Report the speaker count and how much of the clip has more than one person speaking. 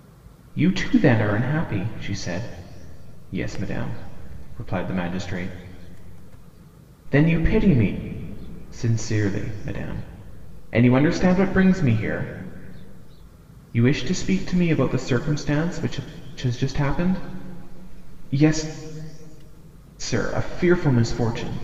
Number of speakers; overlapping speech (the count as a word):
one, no overlap